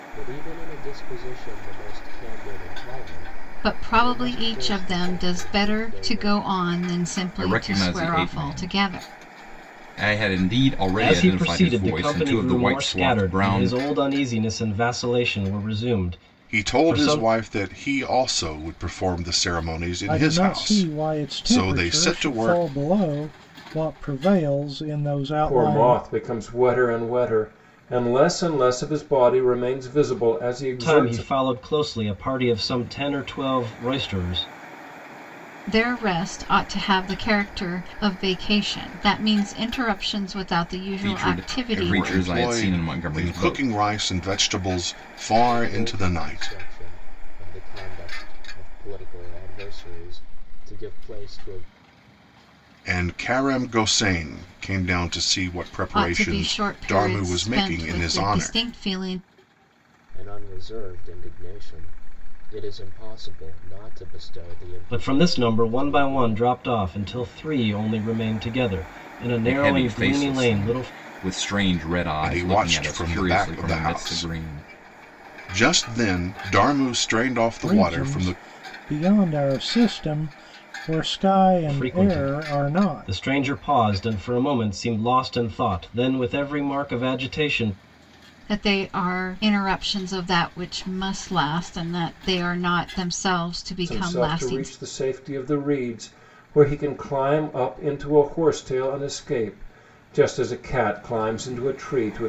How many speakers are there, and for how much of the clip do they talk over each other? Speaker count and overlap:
seven, about 27%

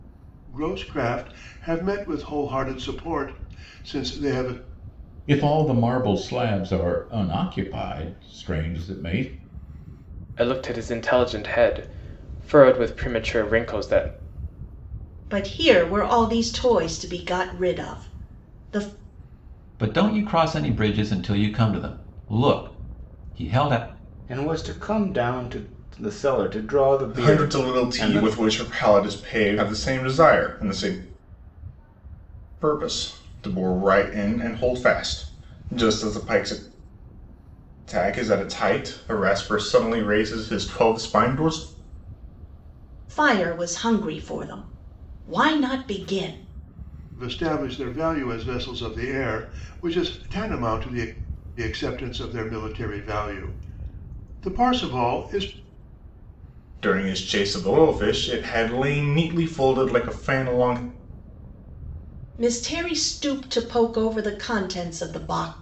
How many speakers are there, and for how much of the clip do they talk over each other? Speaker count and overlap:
seven, about 2%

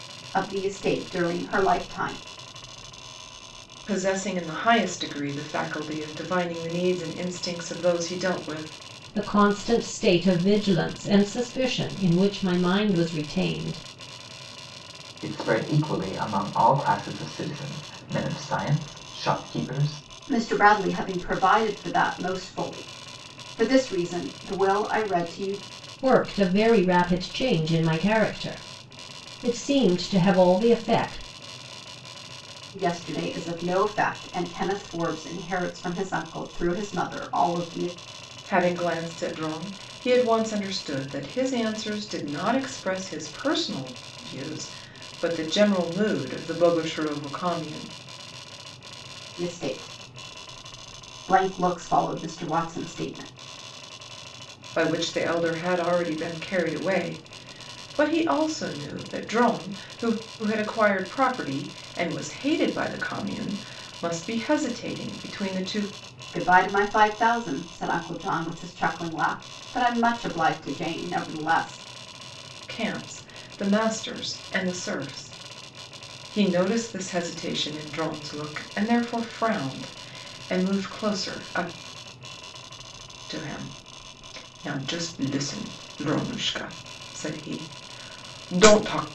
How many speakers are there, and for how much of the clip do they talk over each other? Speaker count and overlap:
four, no overlap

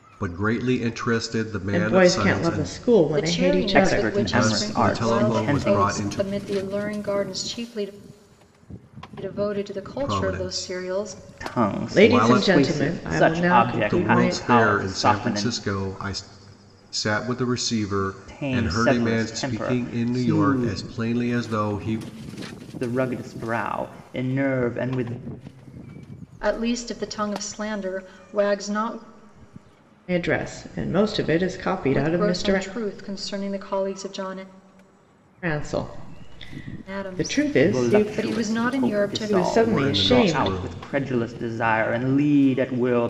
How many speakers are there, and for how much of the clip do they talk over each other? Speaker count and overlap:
four, about 40%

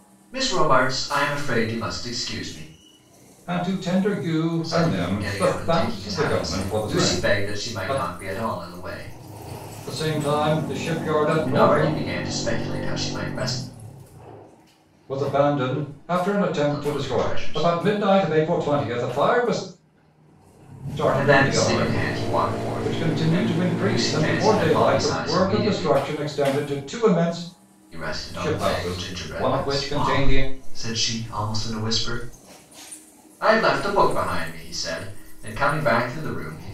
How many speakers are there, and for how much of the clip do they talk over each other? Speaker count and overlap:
two, about 30%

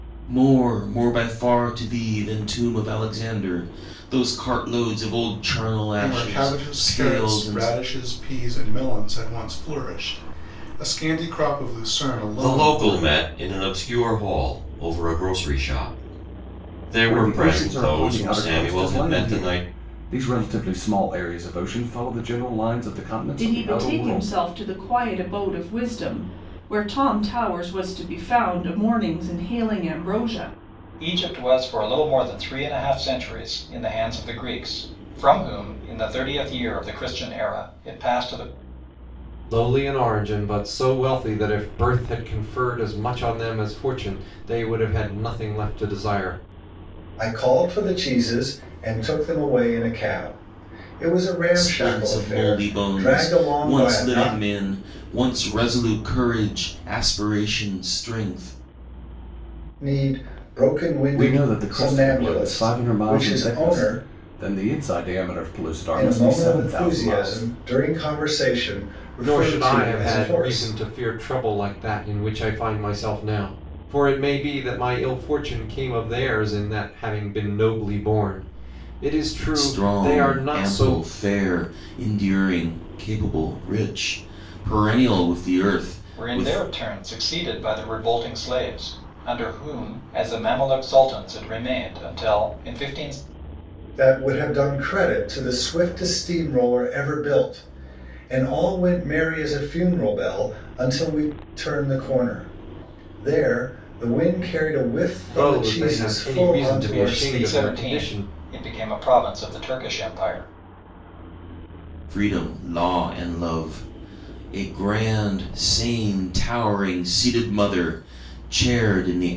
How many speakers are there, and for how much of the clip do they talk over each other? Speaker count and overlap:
eight, about 17%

